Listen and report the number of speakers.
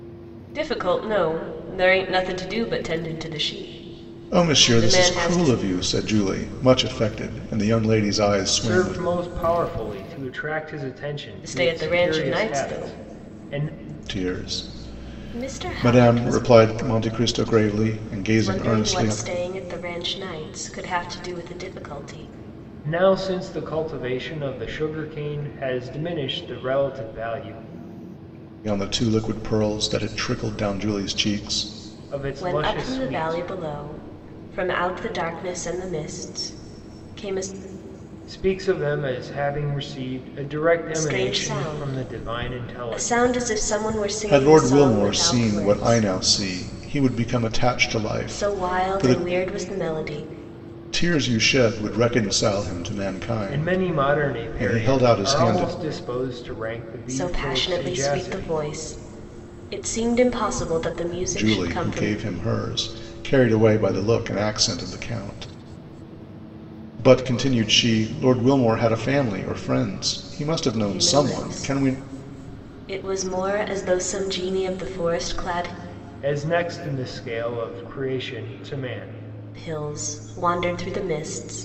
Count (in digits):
3